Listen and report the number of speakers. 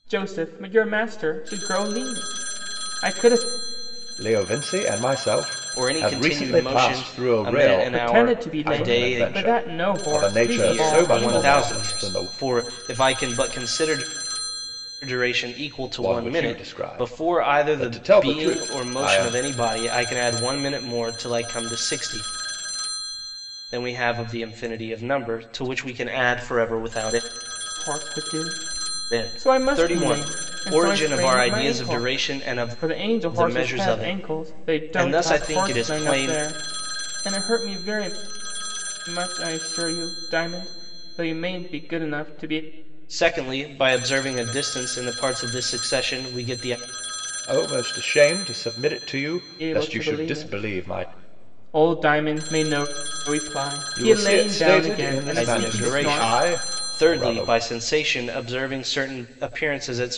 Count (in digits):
3